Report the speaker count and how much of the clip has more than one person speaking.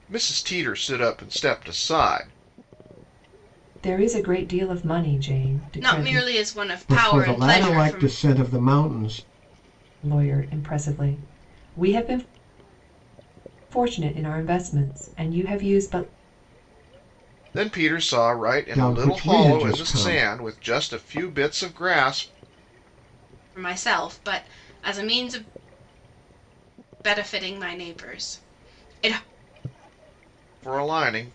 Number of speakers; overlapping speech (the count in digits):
4, about 11%